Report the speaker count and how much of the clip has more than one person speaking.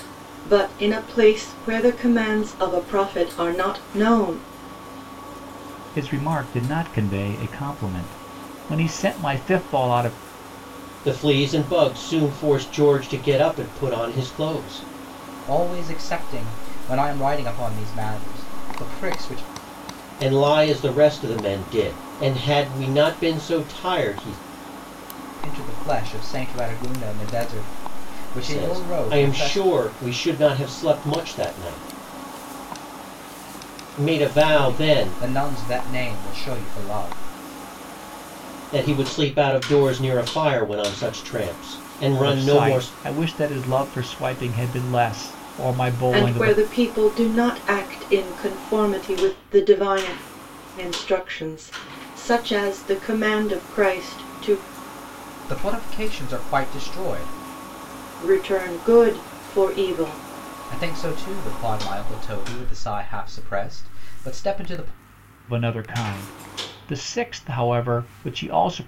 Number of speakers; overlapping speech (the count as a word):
four, about 5%